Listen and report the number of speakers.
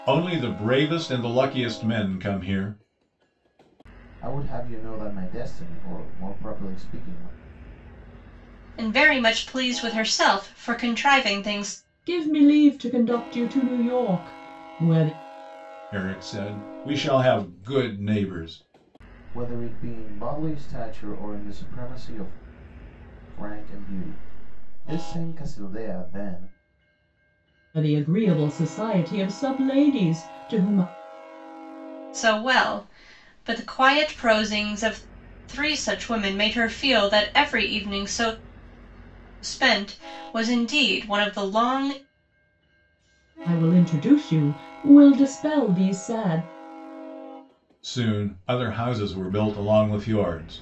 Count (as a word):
four